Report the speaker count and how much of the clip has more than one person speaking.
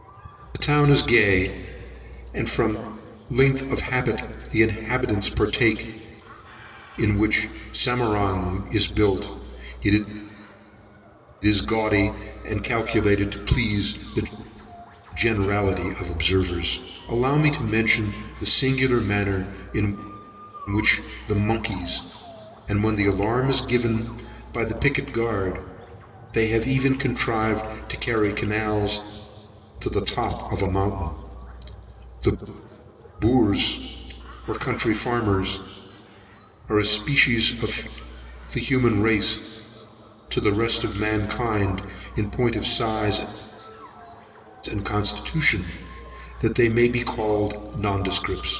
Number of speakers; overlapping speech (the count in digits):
1, no overlap